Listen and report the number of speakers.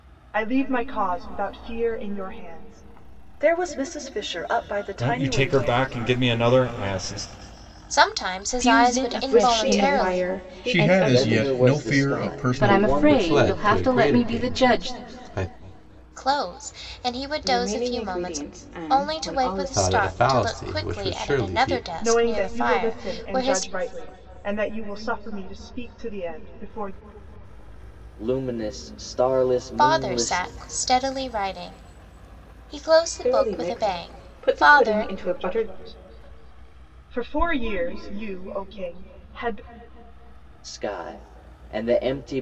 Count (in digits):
10